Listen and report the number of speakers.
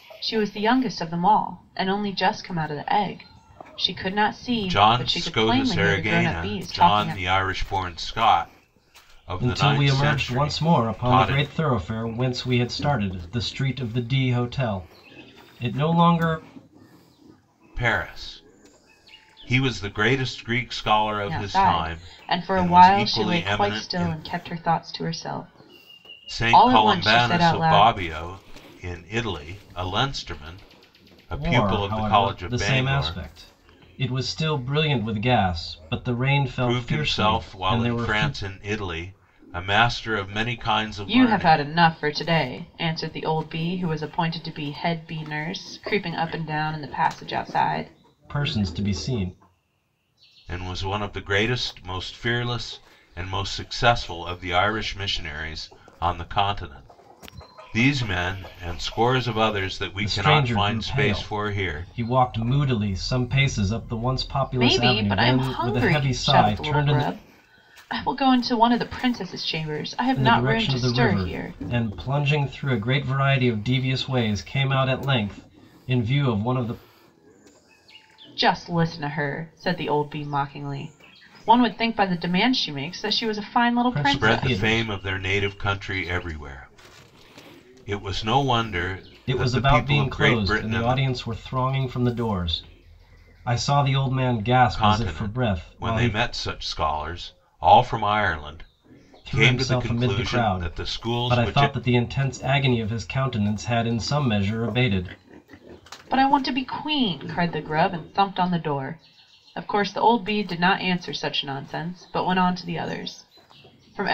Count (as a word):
three